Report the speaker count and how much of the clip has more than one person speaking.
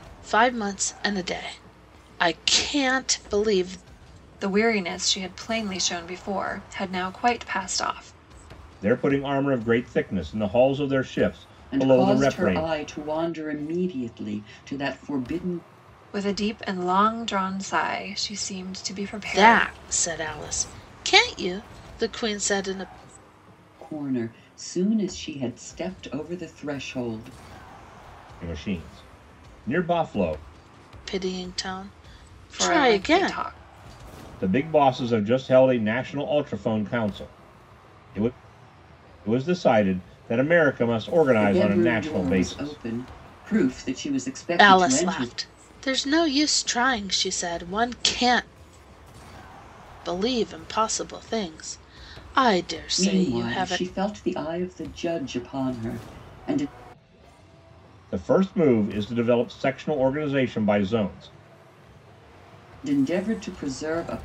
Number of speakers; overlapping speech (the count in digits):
4, about 9%